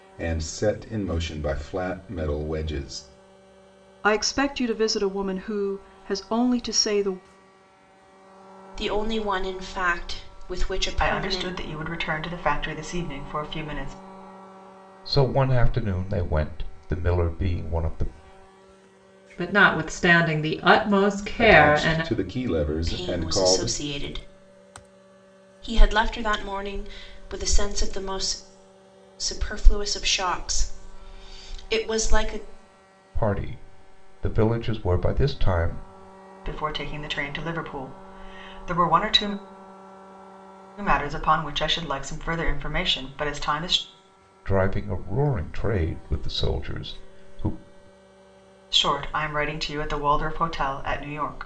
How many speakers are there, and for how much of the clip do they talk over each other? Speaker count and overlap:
six, about 4%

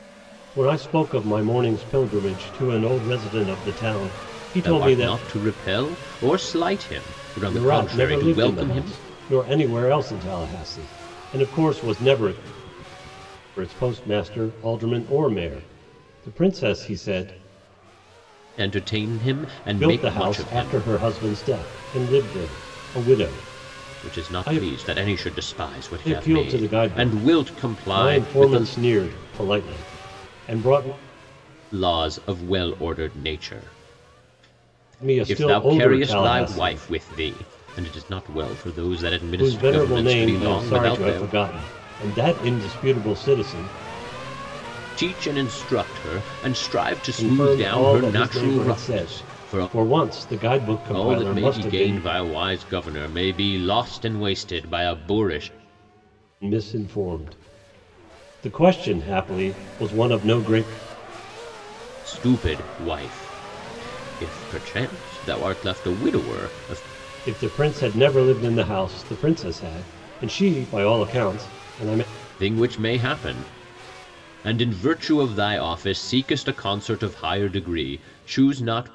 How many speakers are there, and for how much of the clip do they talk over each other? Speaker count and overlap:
two, about 18%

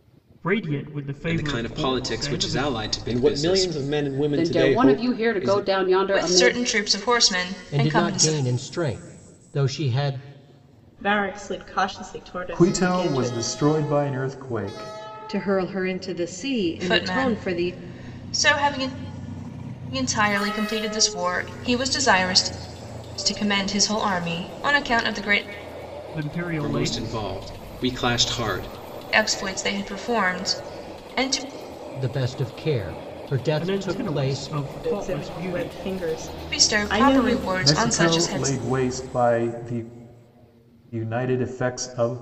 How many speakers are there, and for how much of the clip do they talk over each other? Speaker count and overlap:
nine, about 26%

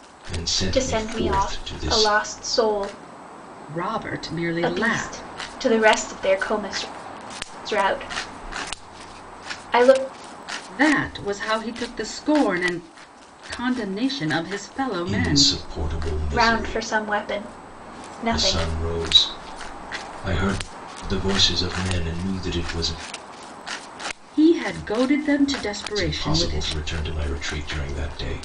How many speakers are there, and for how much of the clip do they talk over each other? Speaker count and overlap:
three, about 15%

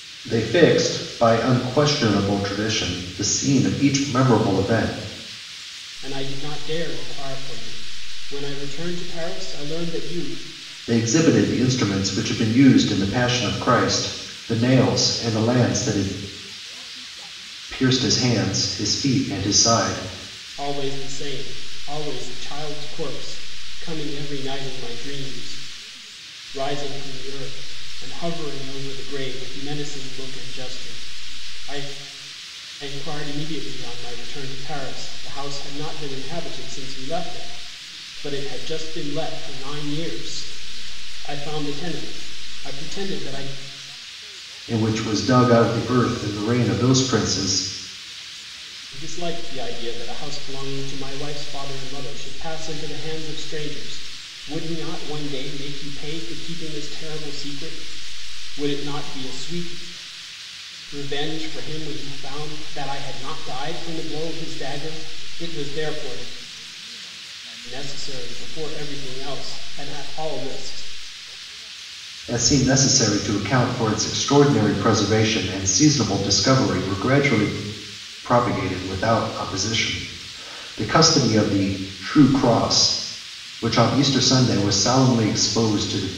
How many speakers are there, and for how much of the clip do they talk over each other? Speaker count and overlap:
two, no overlap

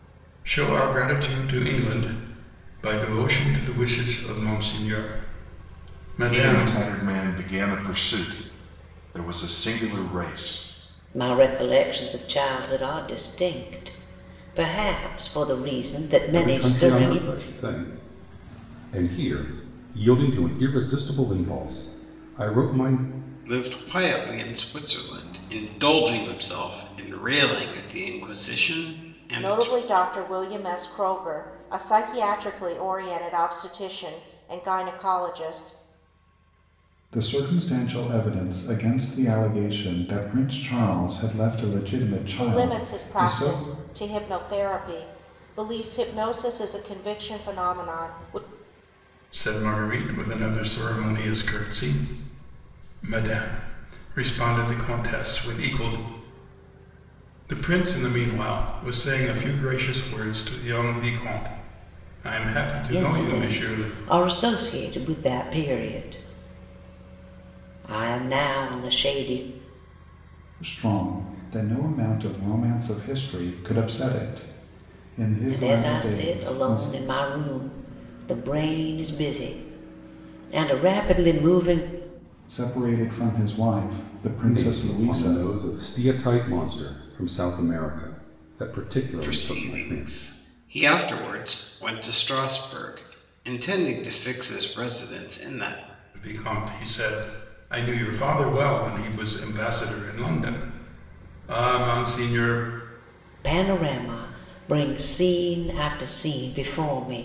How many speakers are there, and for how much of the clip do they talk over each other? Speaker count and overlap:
seven, about 7%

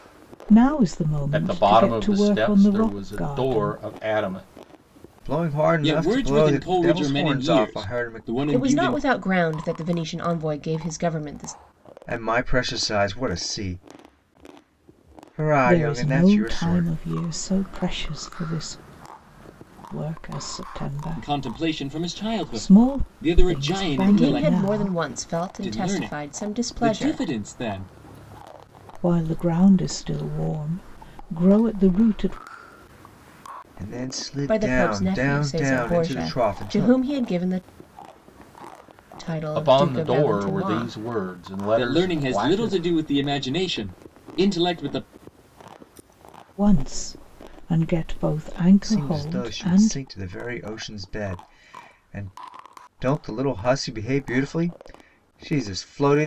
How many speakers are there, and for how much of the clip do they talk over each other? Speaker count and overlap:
five, about 33%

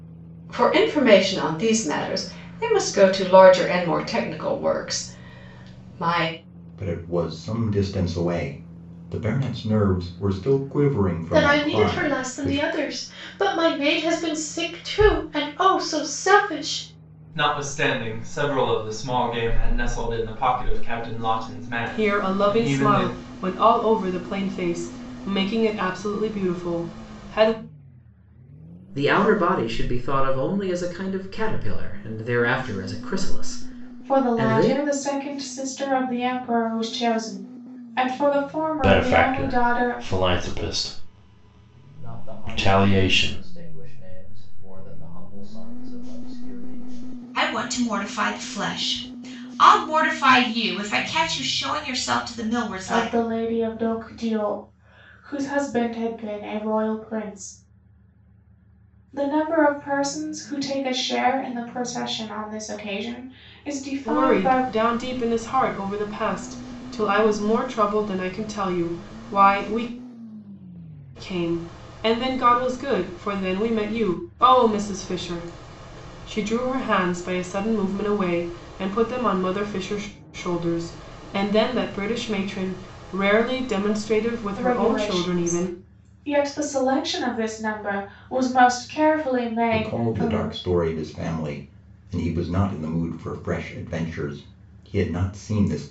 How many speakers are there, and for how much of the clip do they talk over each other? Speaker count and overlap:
ten, about 9%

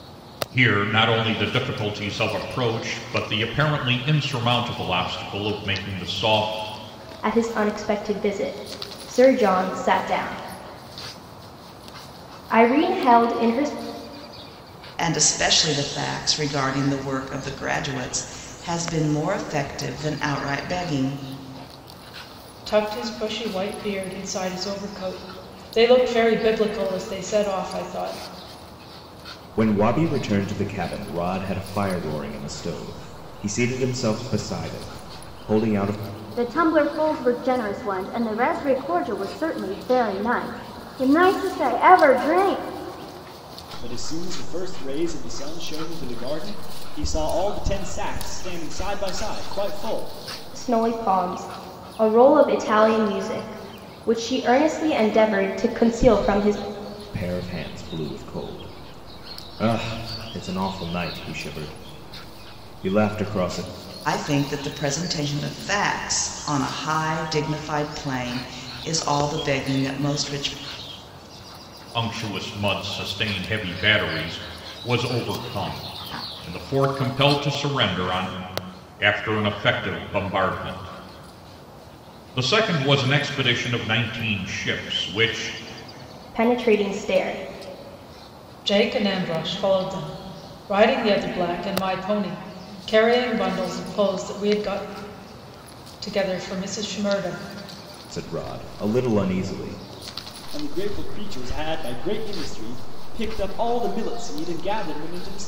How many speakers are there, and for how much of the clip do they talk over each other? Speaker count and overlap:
seven, no overlap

